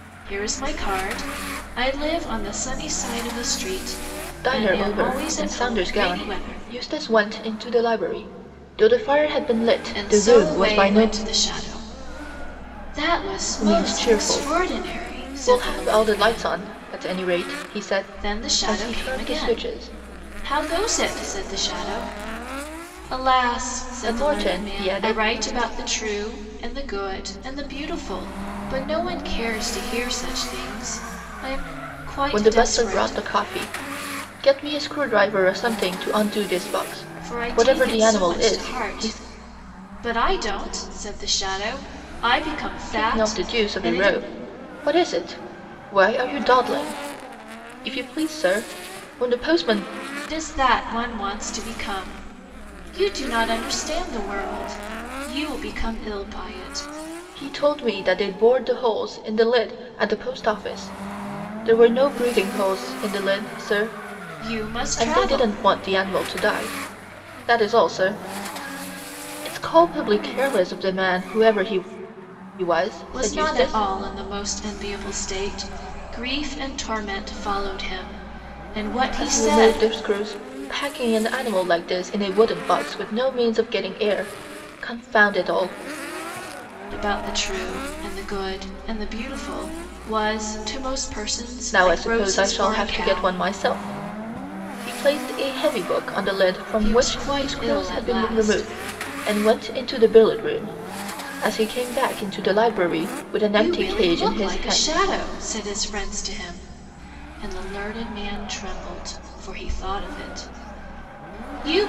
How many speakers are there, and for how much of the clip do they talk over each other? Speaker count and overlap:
two, about 19%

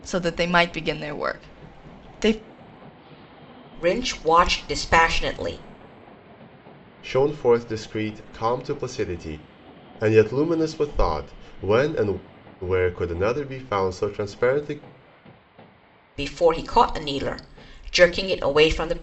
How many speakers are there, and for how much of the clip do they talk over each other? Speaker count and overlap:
three, no overlap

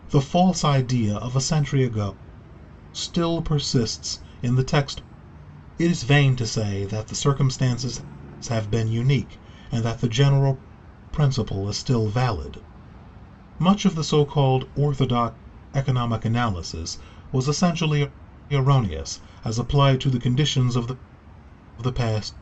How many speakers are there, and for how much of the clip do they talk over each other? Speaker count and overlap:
one, no overlap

